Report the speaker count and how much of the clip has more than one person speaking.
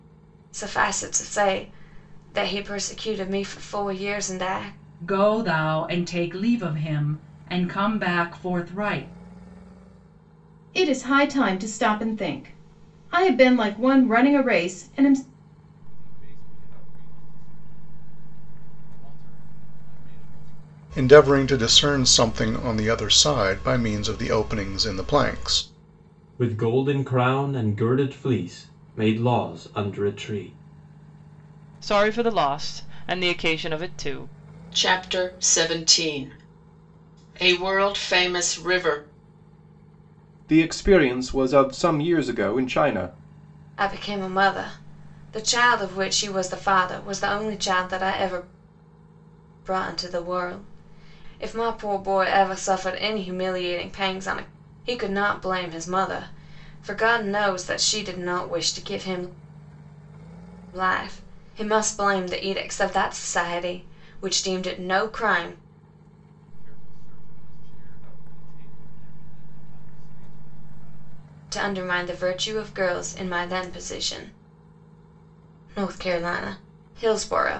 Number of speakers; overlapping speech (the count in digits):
9, no overlap